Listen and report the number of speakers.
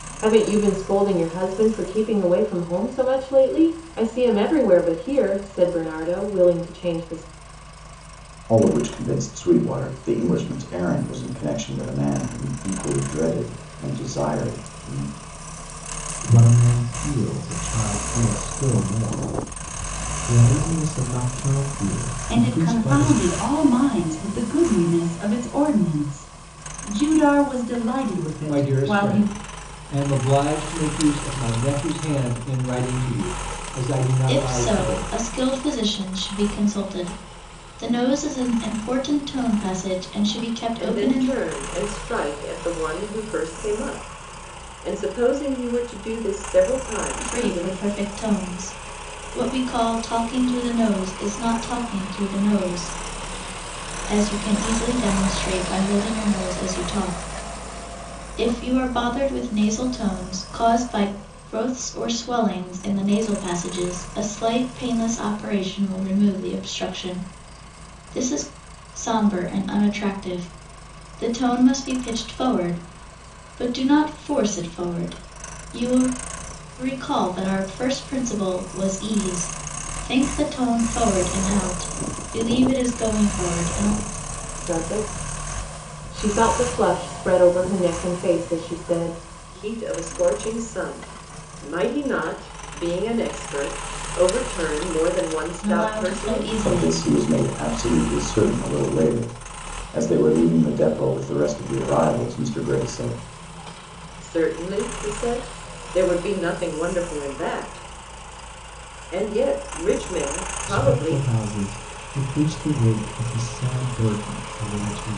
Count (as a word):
seven